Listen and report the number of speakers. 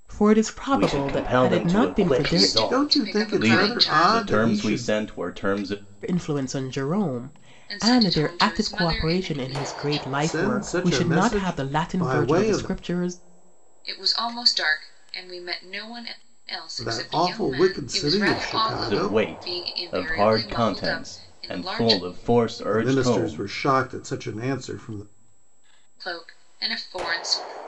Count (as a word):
four